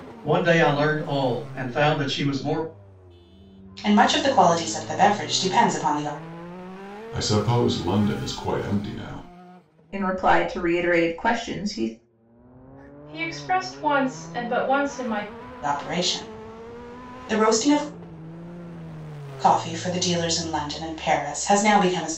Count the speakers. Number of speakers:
five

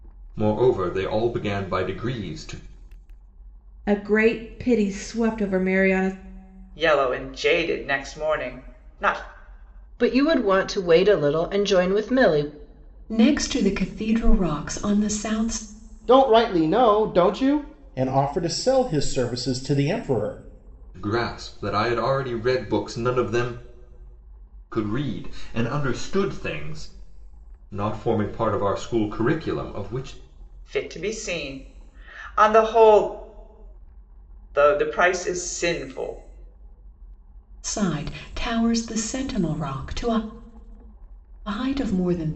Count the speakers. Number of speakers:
seven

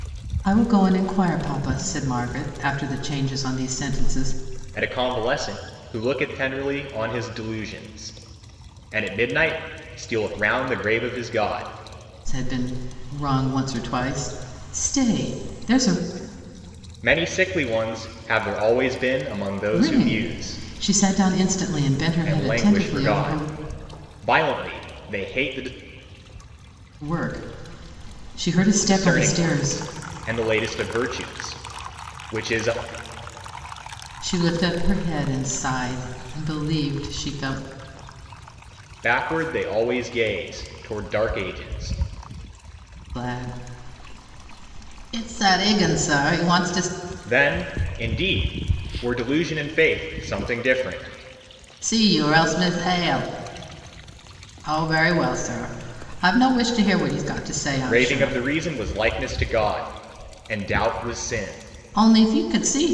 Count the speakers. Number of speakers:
two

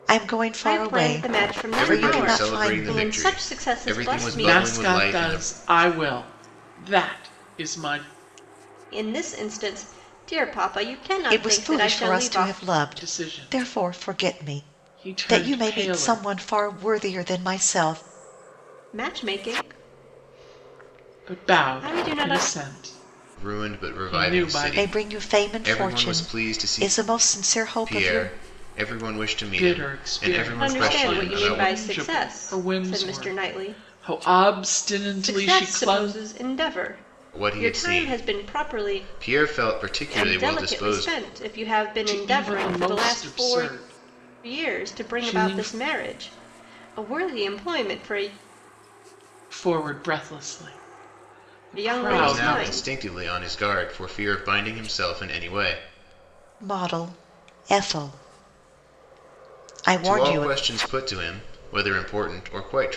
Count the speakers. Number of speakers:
four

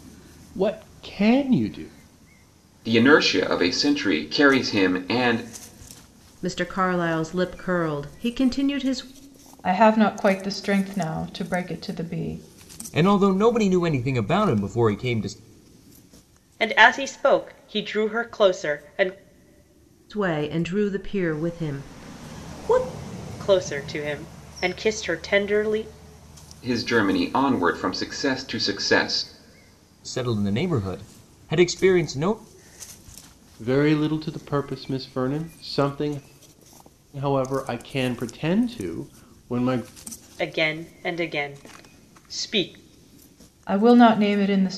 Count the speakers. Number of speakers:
six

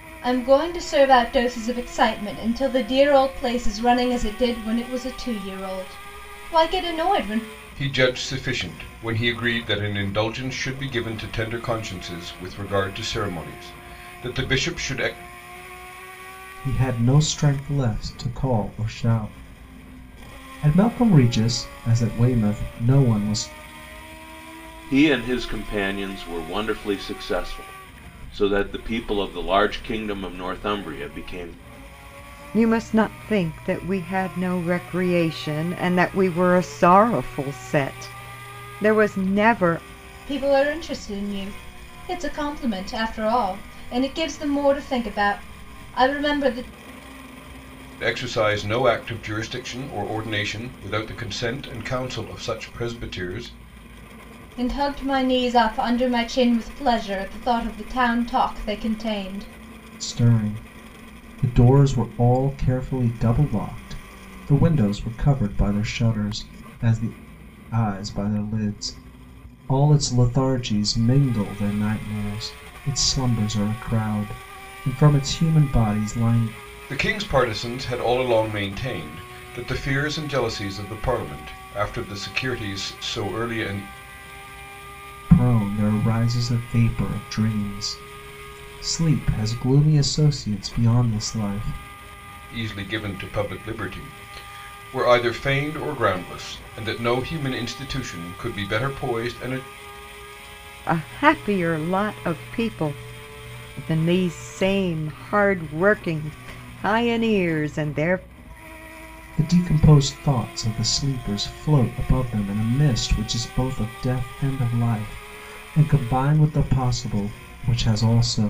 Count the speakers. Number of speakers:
five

